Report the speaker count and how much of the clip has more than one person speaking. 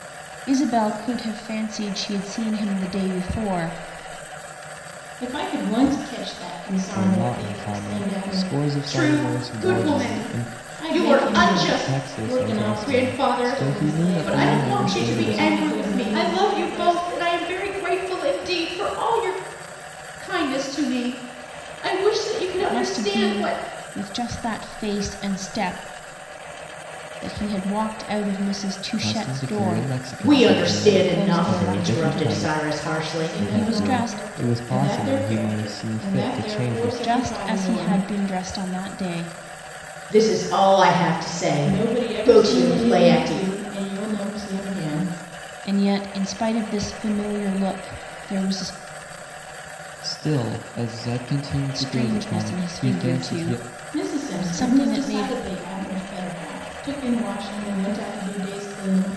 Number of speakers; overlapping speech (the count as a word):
four, about 43%